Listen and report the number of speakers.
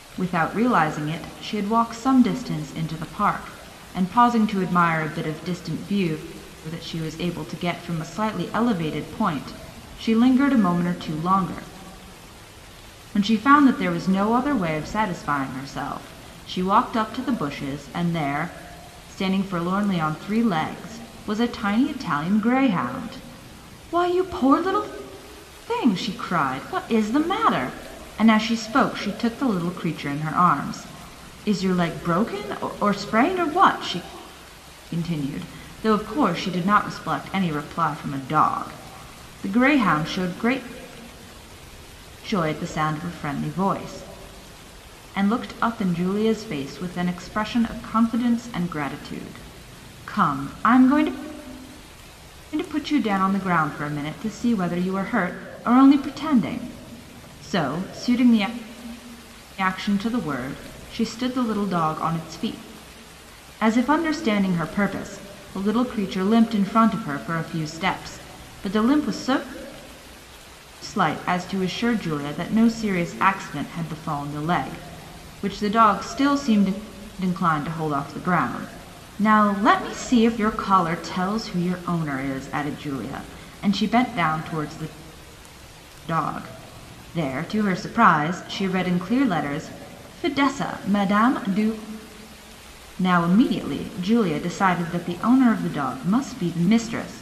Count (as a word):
one